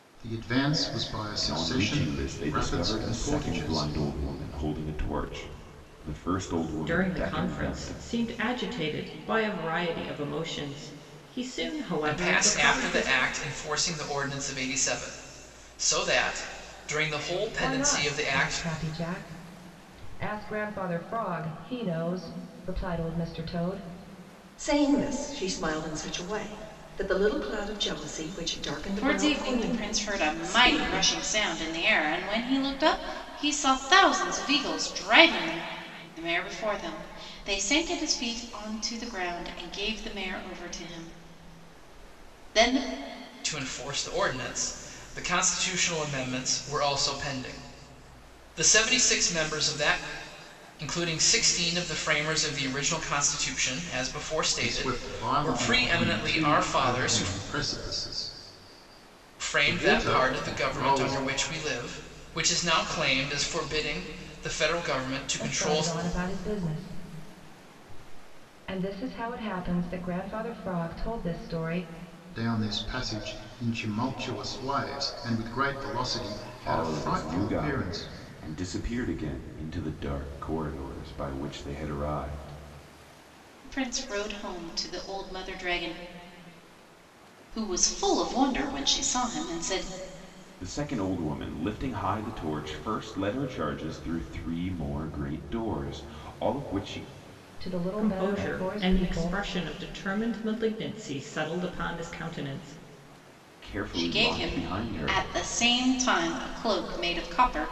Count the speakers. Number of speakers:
7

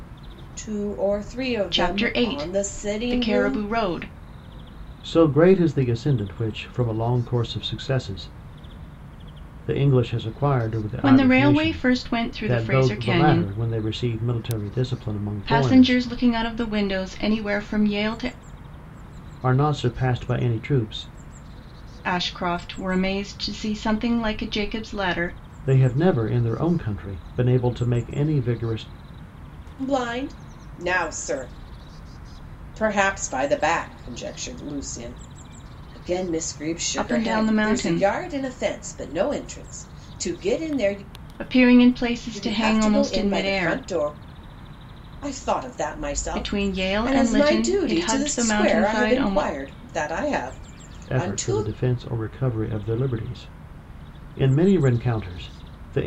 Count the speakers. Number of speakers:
3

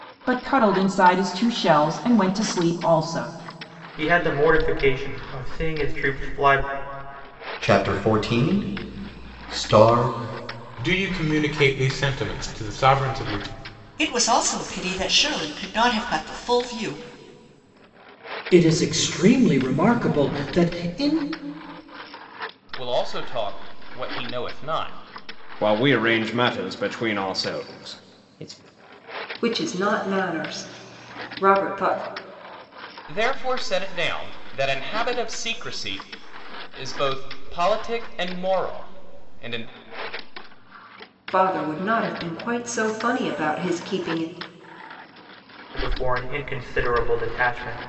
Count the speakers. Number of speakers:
9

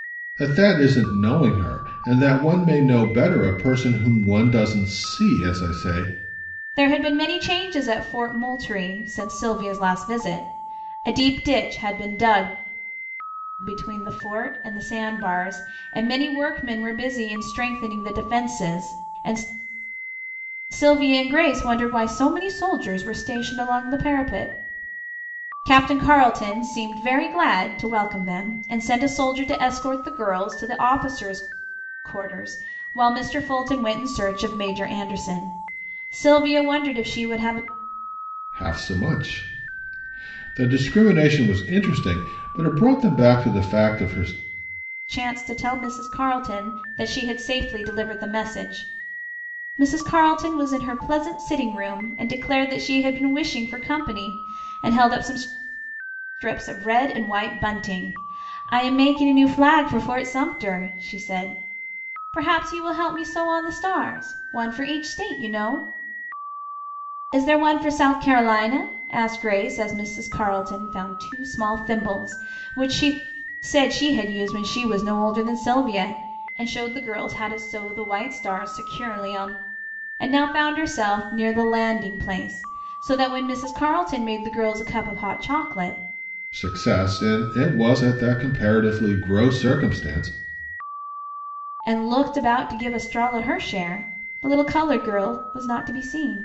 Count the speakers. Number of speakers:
2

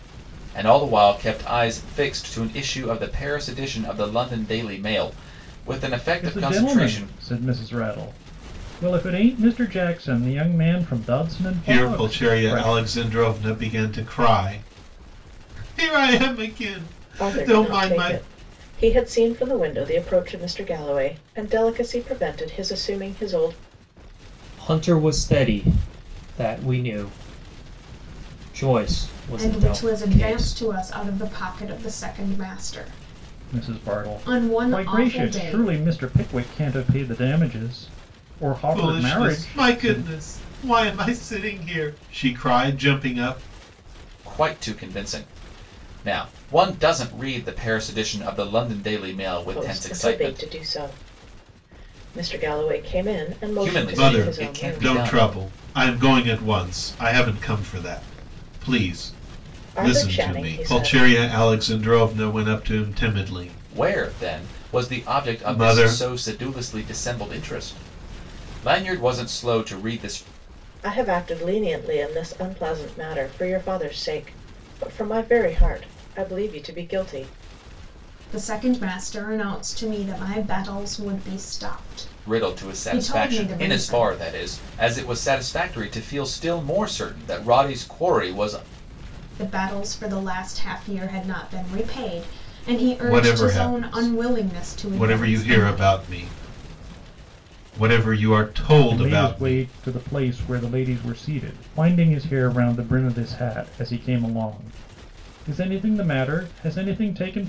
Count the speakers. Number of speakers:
6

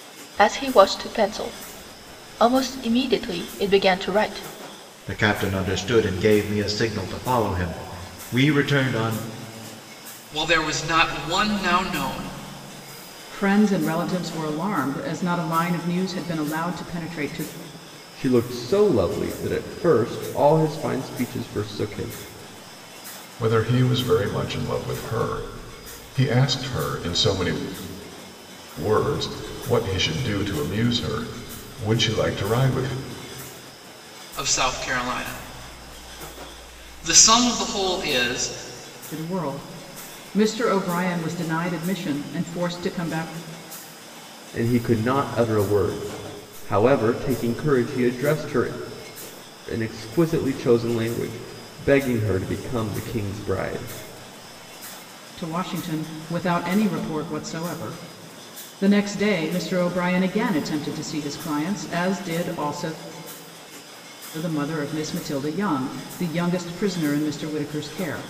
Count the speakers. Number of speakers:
6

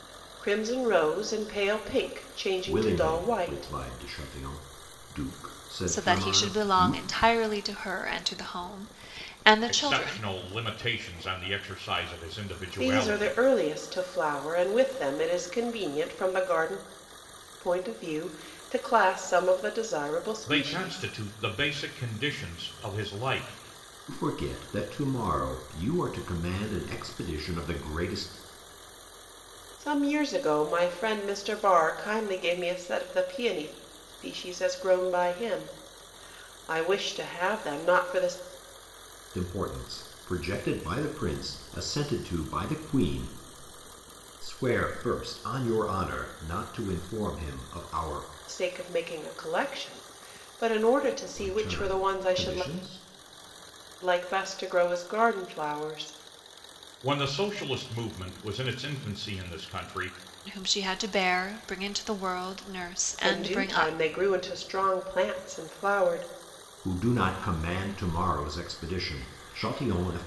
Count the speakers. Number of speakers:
4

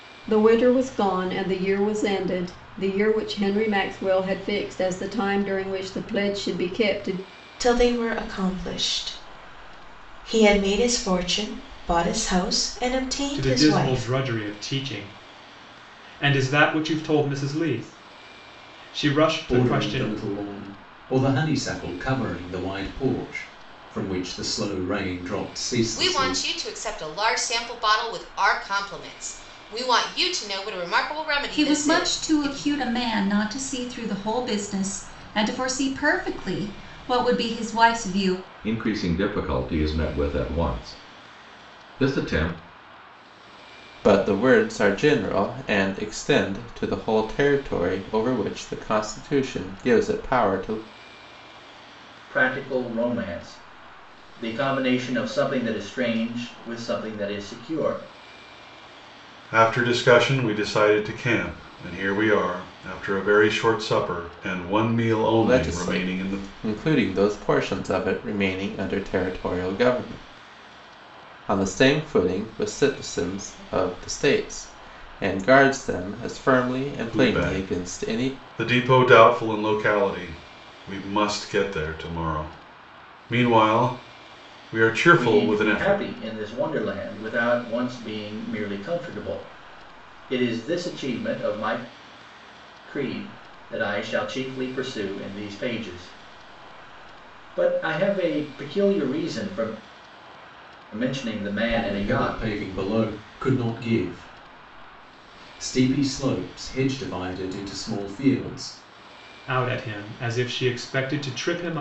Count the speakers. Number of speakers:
10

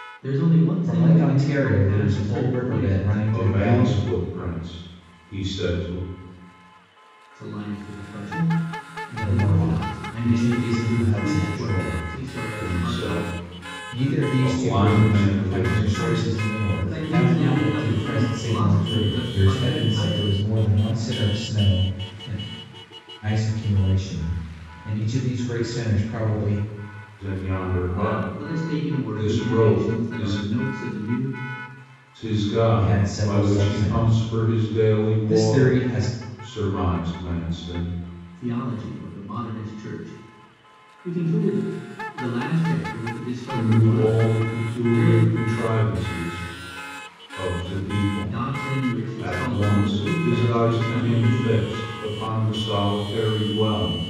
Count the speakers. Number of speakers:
3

